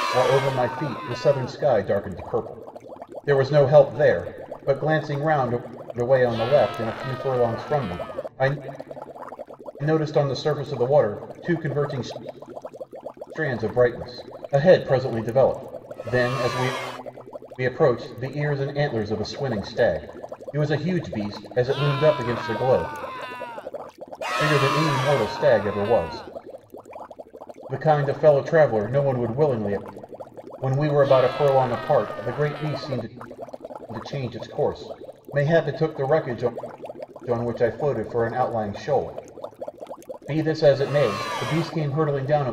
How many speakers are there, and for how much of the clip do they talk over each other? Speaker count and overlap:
one, no overlap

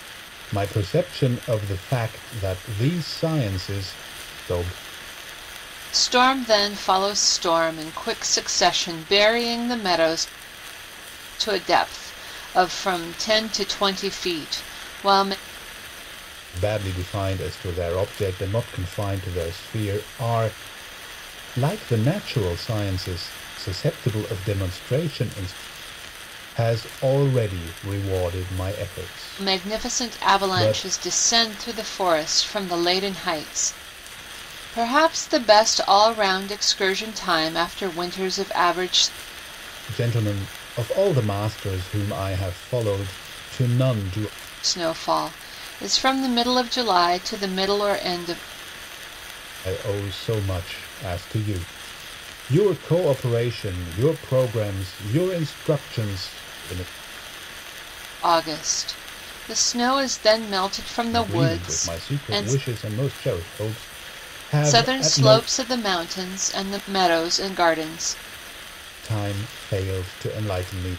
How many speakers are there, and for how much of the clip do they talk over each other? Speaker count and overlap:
two, about 5%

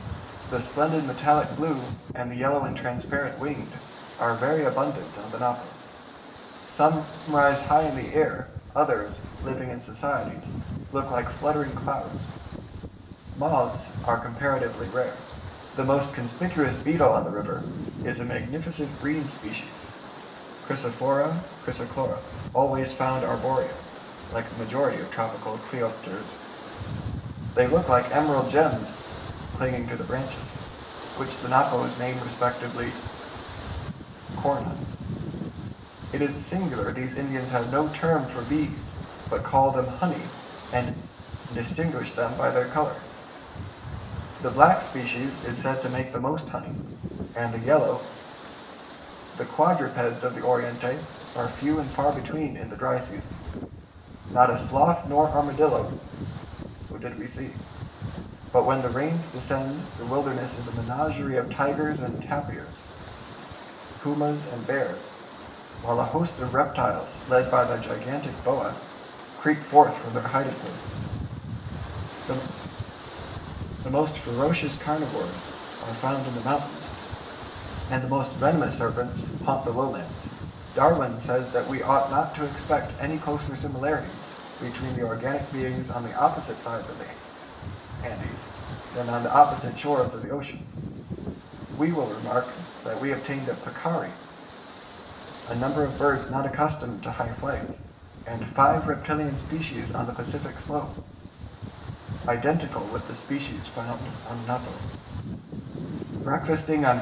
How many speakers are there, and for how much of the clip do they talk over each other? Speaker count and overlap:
one, no overlap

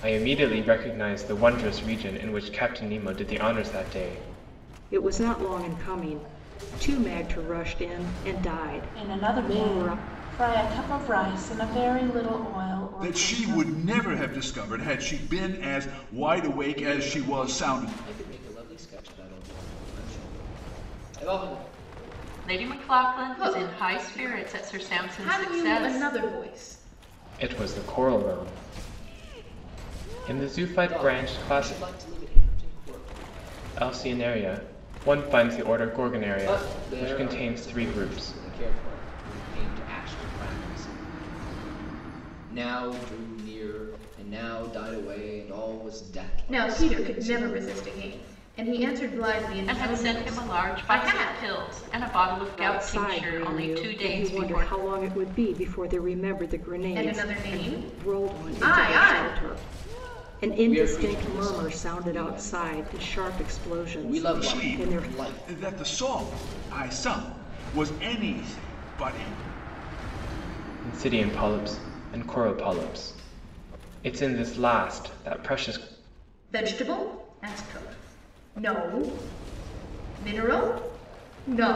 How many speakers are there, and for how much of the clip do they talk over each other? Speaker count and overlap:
seven, about 25%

